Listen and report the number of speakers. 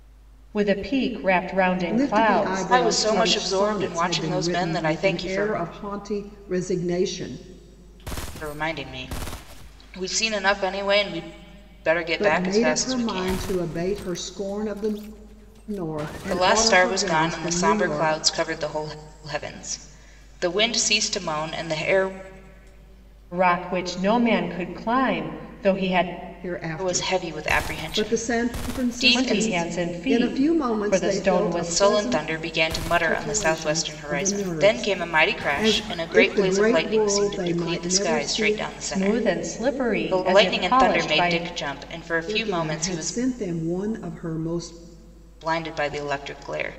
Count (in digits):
3